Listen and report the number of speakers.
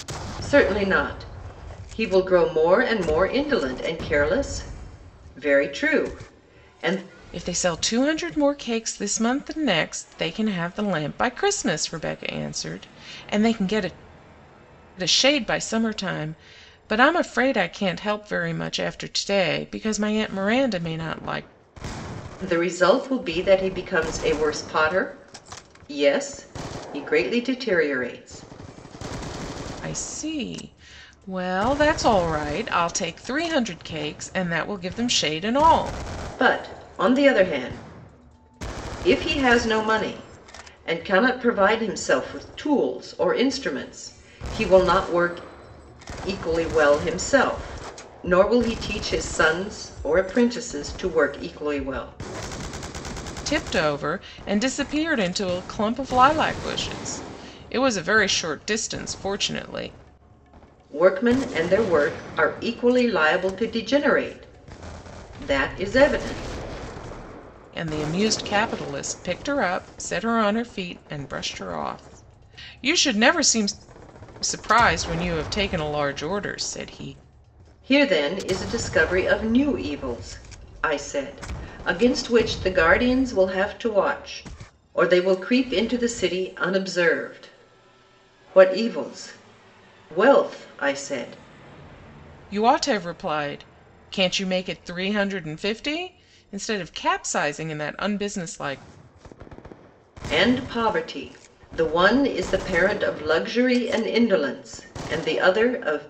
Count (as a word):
two